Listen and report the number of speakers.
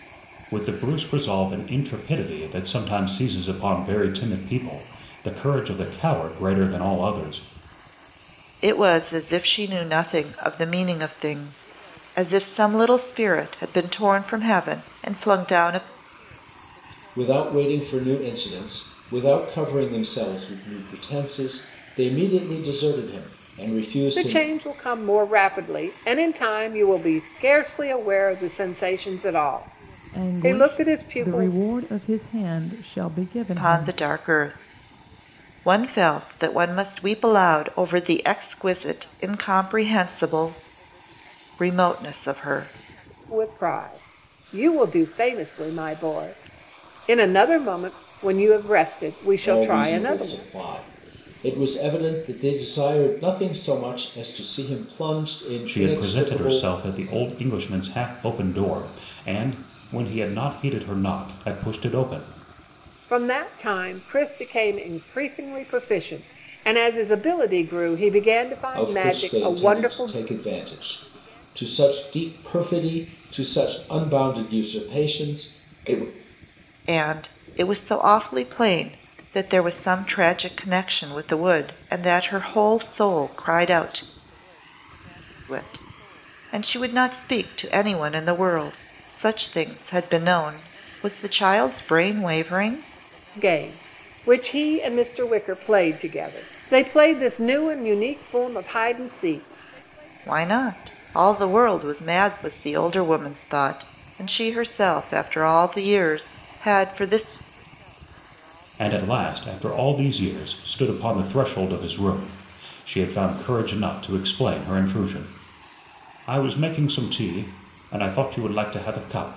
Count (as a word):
five